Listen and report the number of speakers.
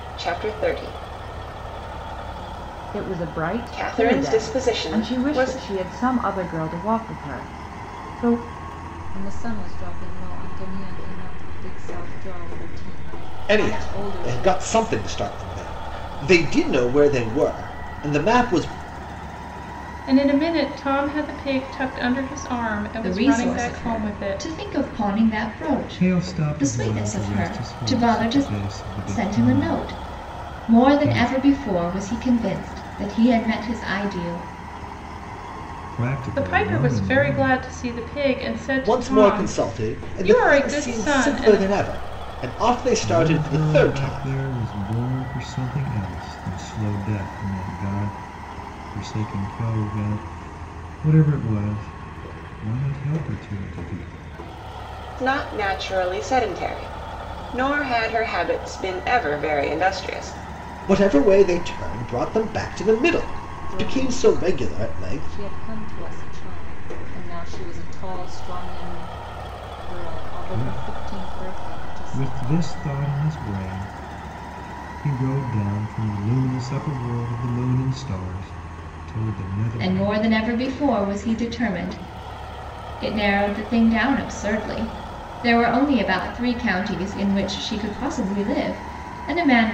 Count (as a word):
seven